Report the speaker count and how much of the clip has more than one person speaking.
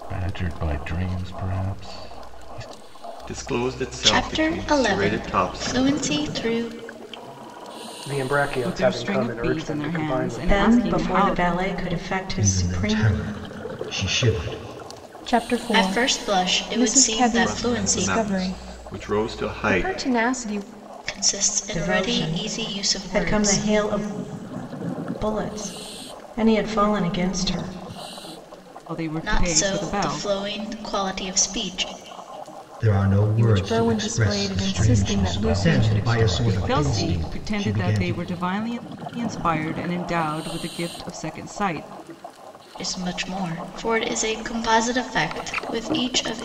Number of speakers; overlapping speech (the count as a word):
eight, about 38%